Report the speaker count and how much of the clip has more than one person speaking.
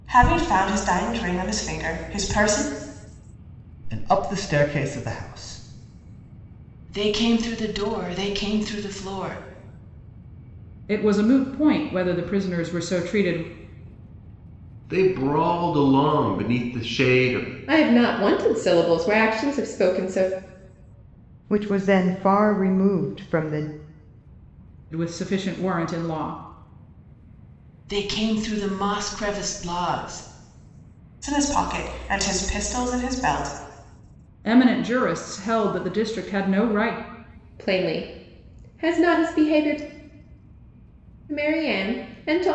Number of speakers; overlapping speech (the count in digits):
7, no overlap